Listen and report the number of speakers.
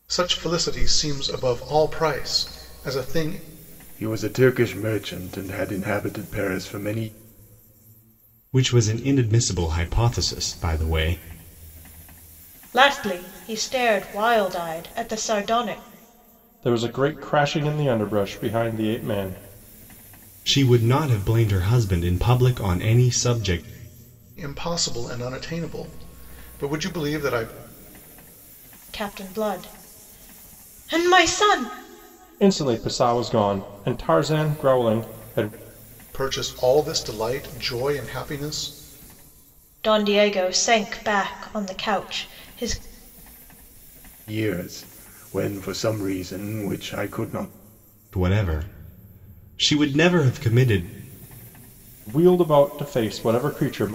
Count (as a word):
five